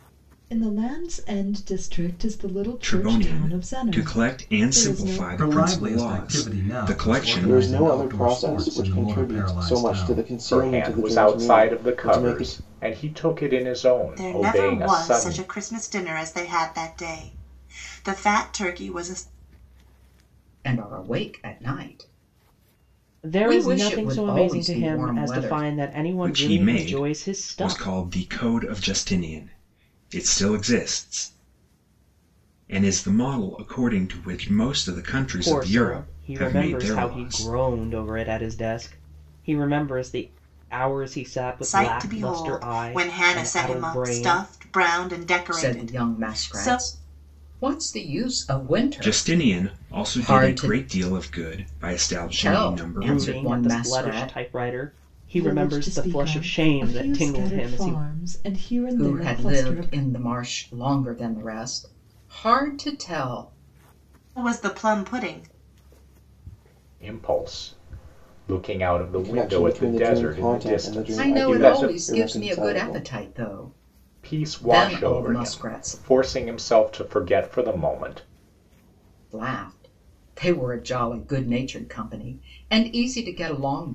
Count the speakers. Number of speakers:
eight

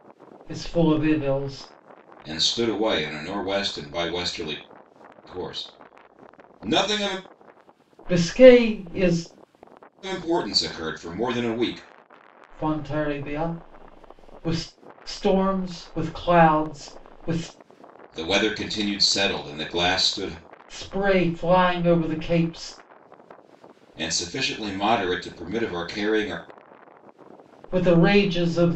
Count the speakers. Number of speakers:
two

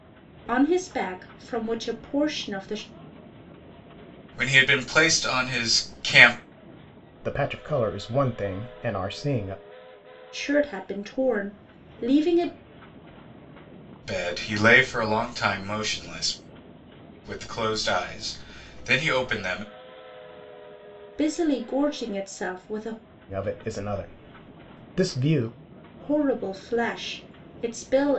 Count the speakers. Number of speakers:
three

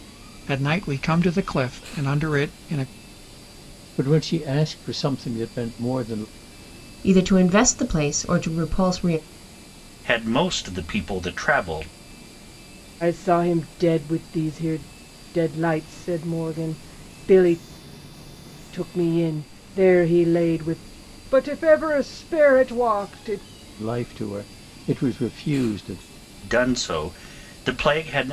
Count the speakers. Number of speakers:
five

